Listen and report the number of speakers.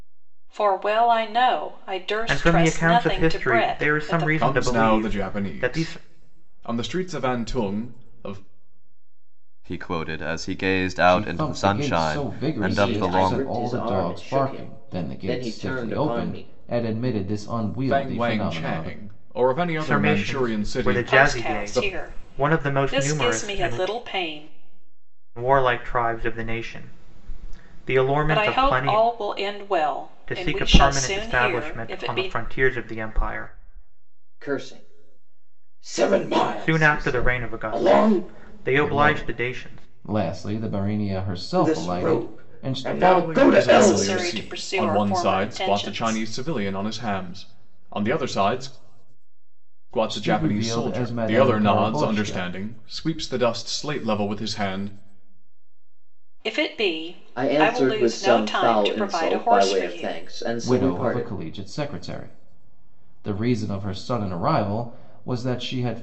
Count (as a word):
six